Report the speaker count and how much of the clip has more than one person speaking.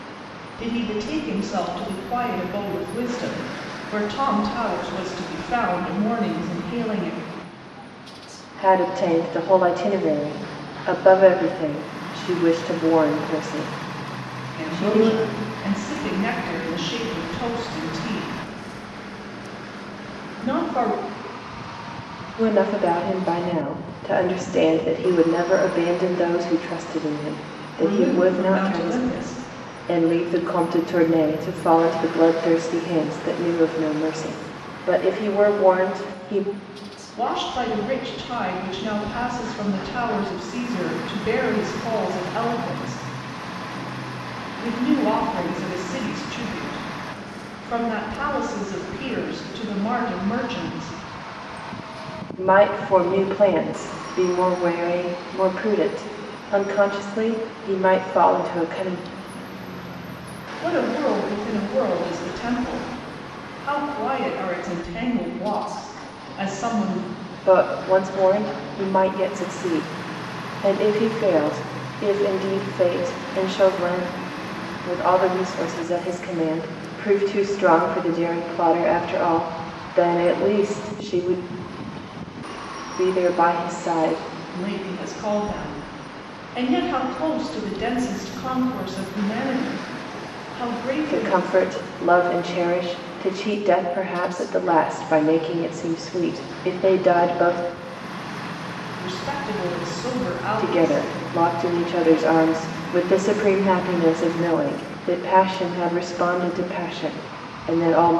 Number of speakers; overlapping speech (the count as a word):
two, about 2%